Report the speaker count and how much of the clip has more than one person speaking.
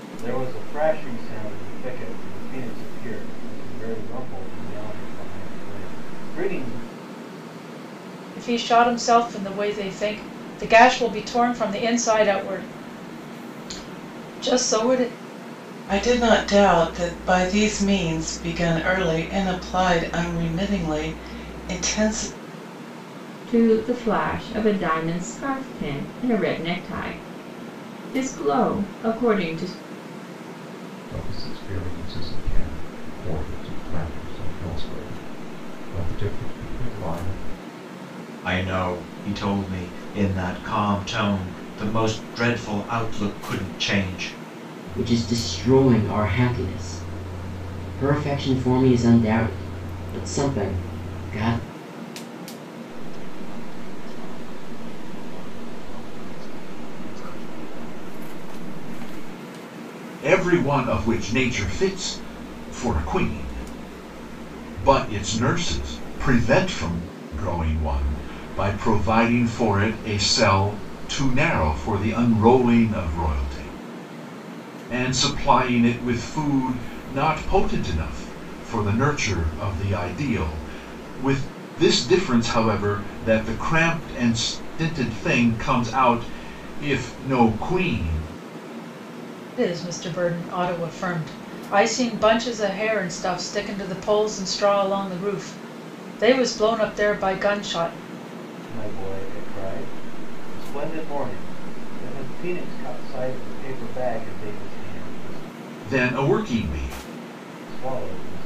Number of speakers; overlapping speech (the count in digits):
9, no overlap